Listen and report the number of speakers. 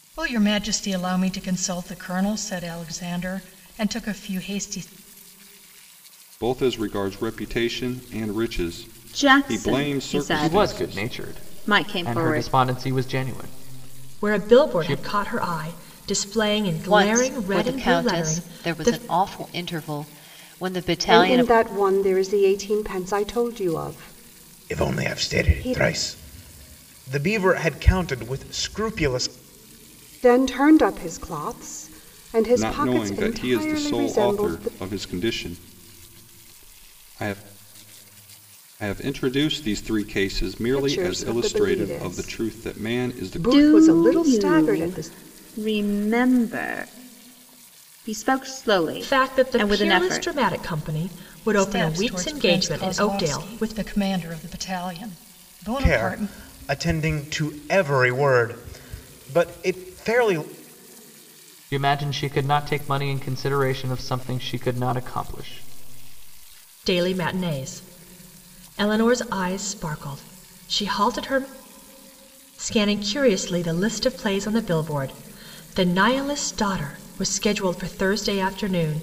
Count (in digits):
8